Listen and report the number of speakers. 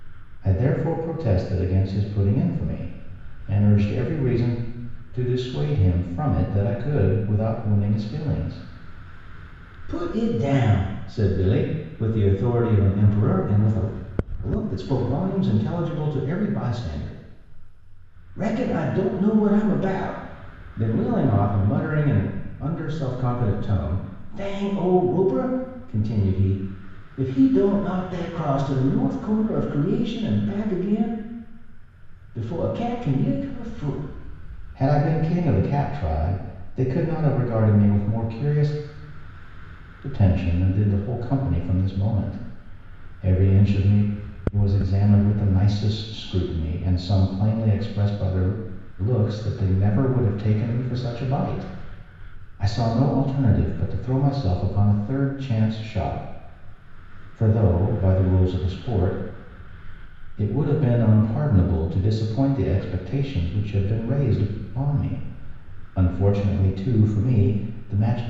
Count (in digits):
1